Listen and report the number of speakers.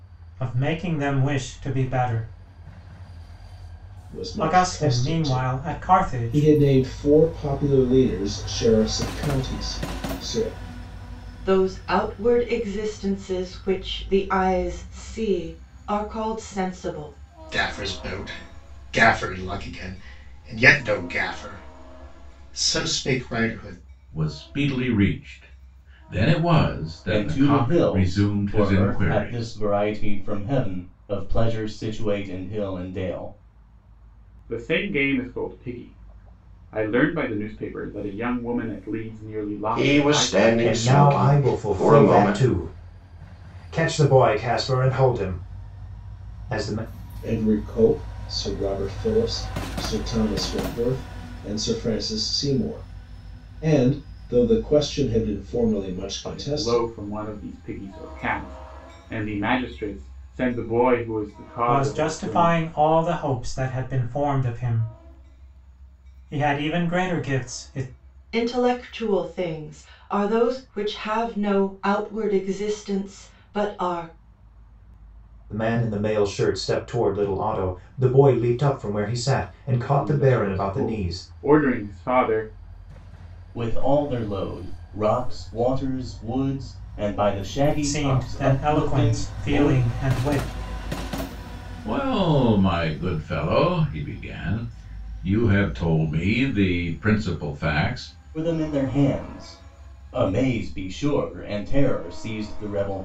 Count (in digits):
9